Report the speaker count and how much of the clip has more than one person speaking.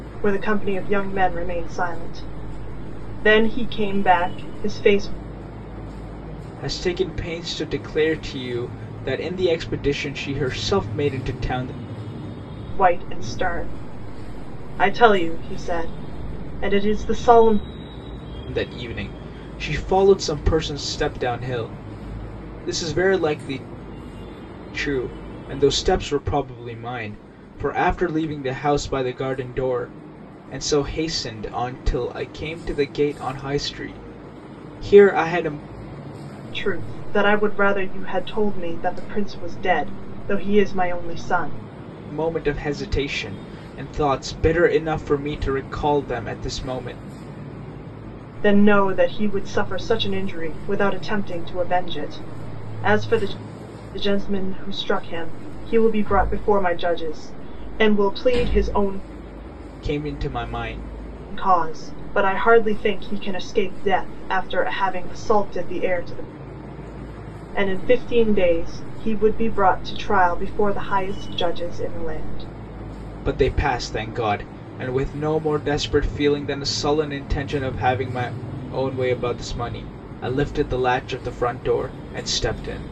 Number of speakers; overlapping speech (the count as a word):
two, no overlap